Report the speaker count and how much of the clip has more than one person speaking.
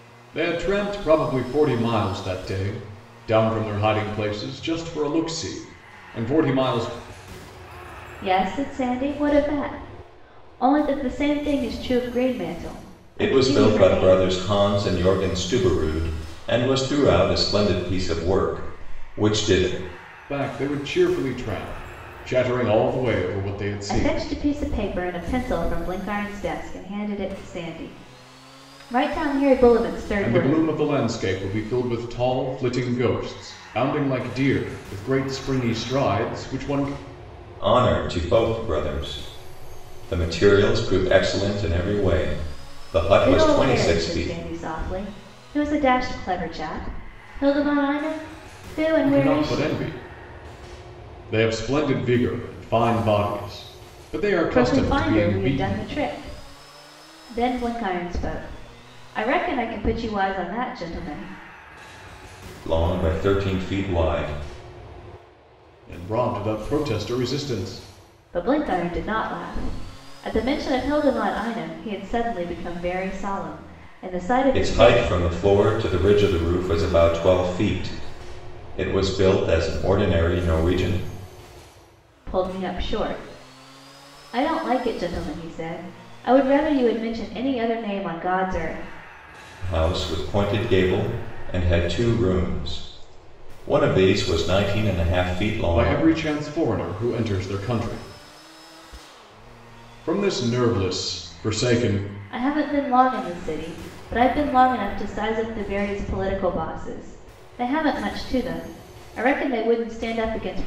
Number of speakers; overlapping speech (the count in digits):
3, about 6%